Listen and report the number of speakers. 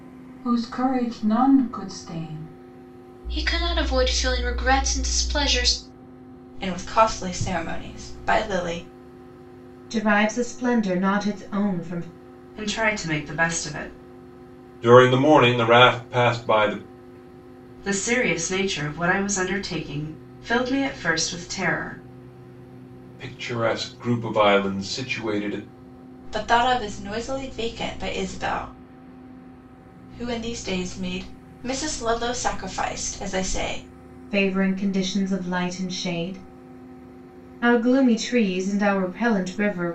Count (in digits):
6